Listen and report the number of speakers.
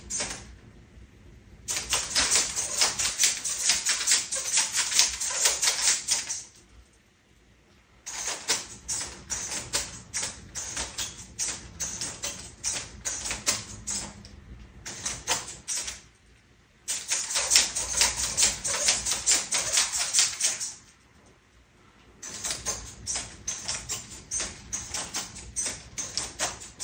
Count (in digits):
0